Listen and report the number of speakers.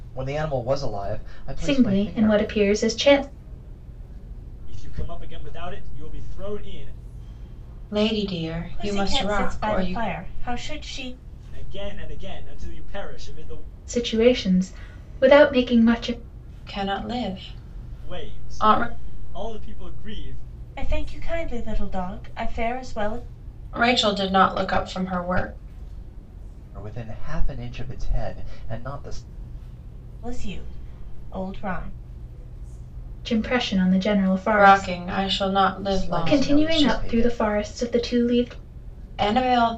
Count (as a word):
five